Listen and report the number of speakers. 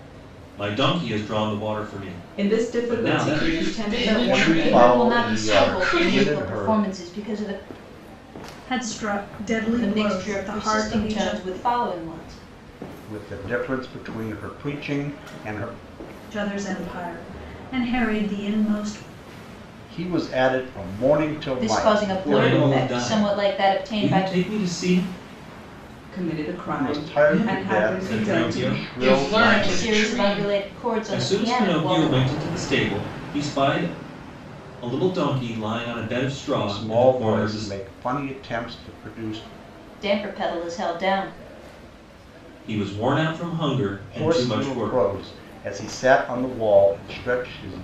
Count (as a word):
six